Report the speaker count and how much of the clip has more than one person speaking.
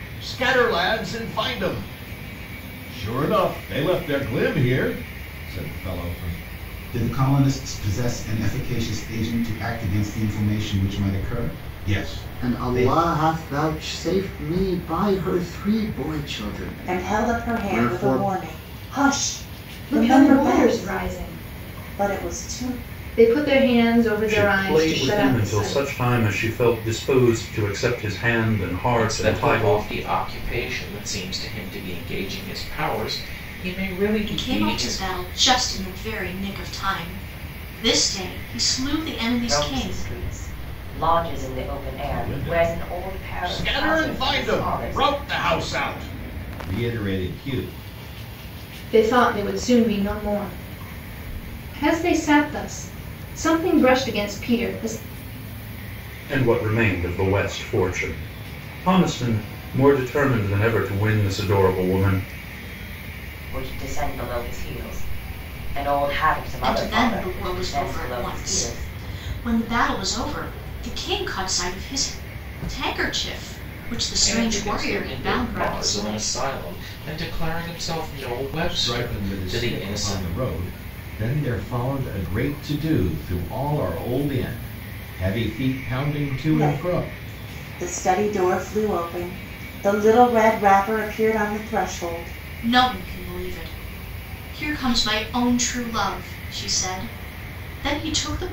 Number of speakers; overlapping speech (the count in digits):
9, about 19%